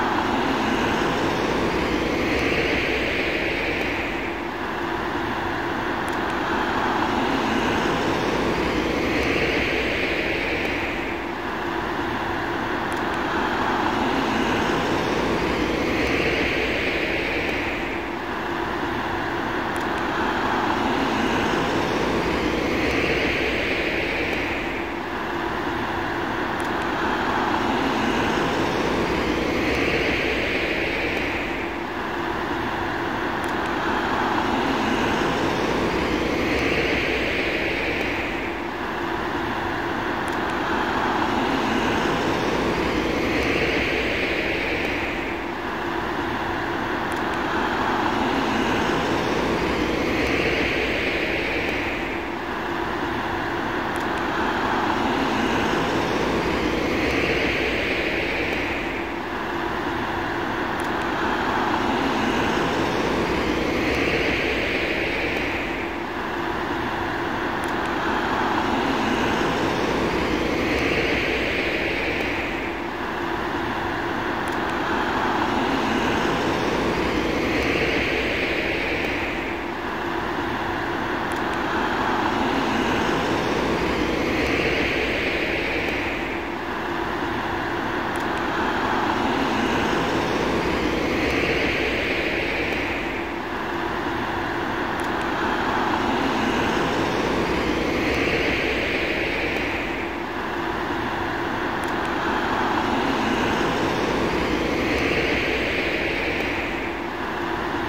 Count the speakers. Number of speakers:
zero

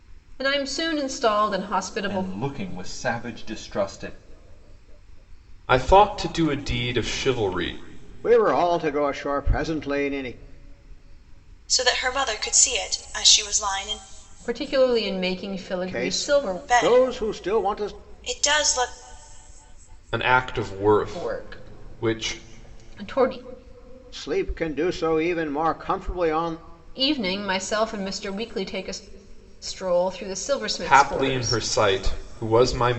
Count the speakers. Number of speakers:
five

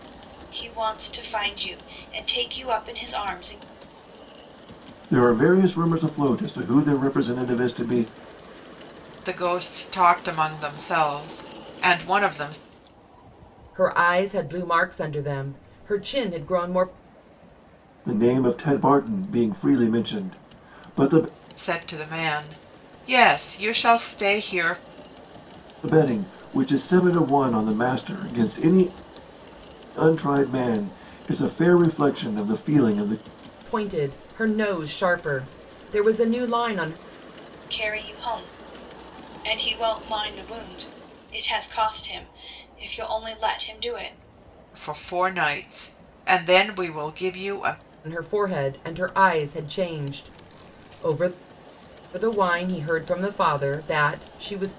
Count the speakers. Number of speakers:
four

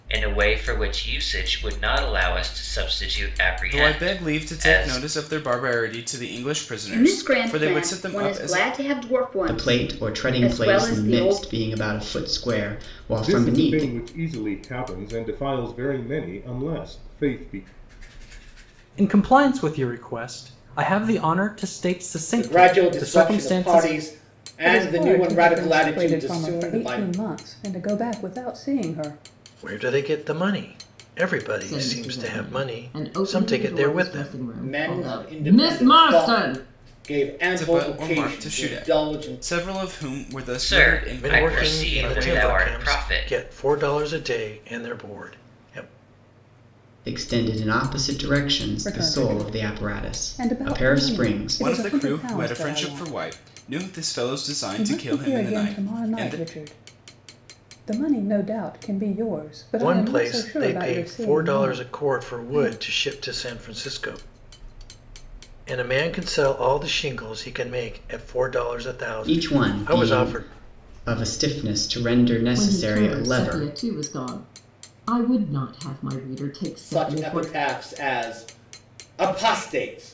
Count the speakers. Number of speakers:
ten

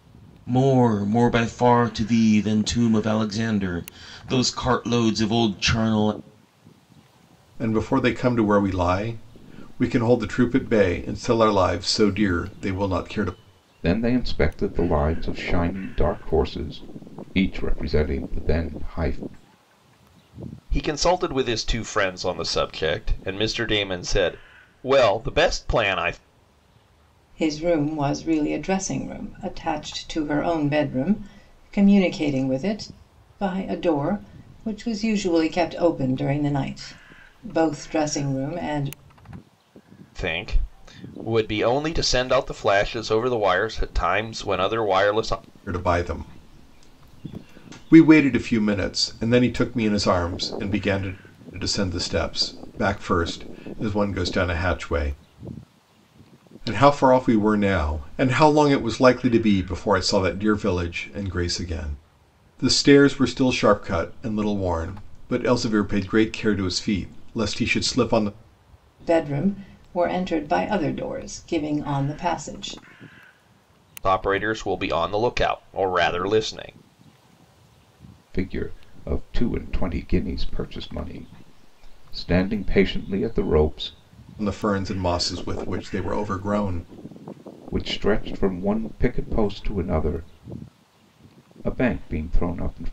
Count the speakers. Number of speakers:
five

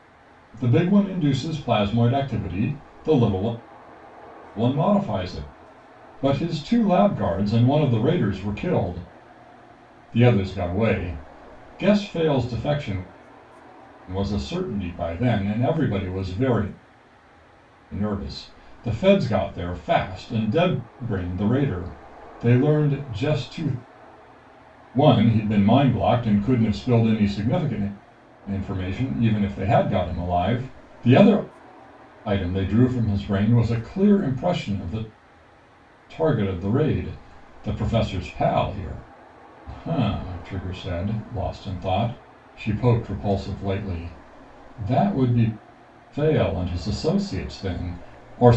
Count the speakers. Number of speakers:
one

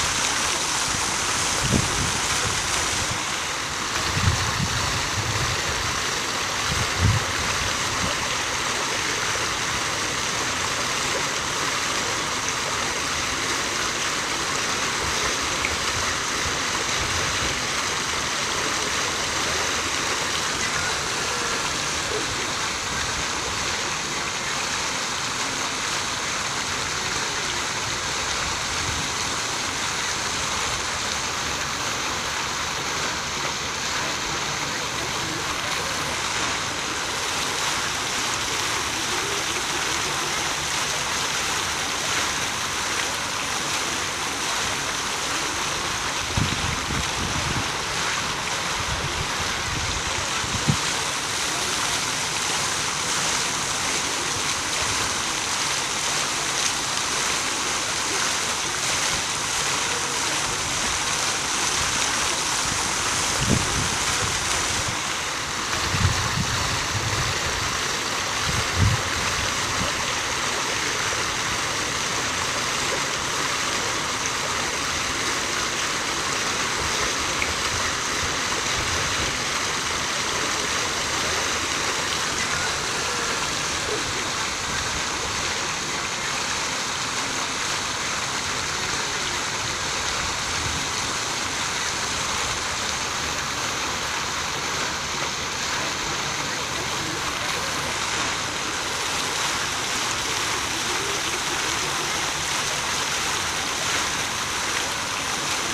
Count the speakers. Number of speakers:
zero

